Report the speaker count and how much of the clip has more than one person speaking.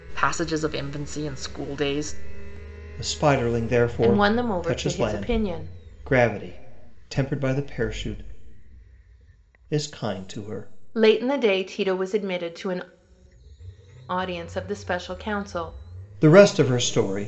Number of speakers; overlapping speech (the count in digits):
3, about 8%